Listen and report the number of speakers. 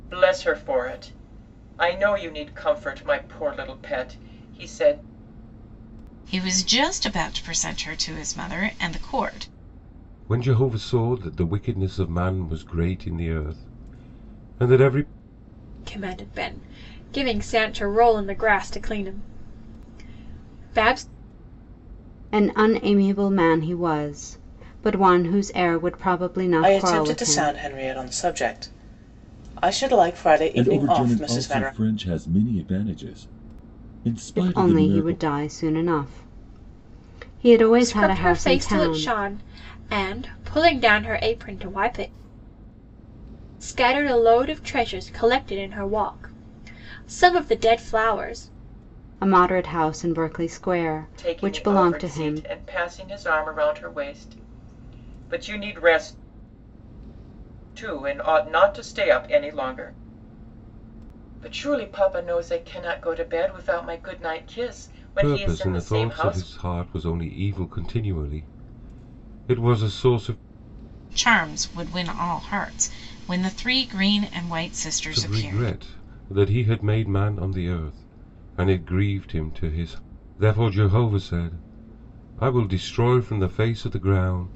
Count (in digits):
7